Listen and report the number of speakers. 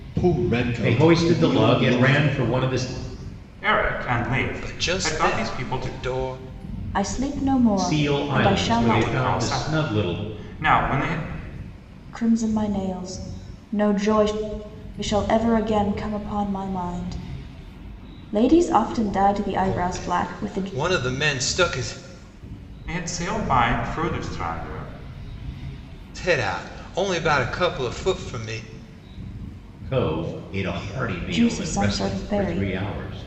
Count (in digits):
5